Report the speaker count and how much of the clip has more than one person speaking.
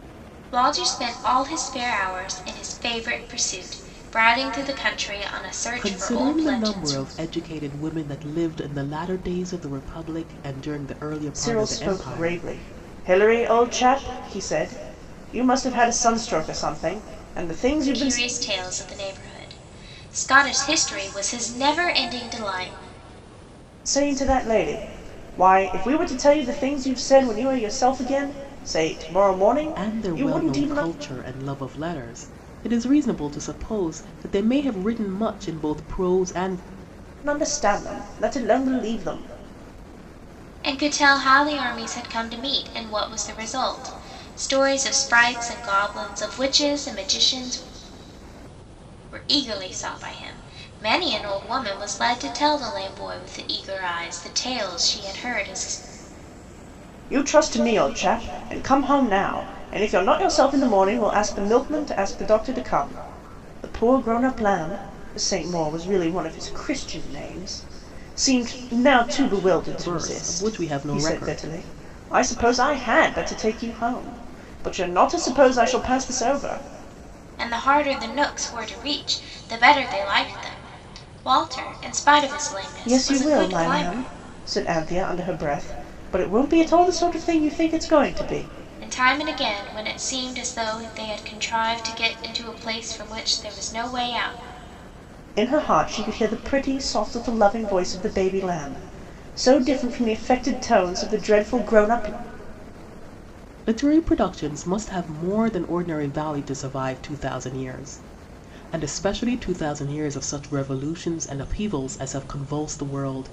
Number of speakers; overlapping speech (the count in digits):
3, about 6%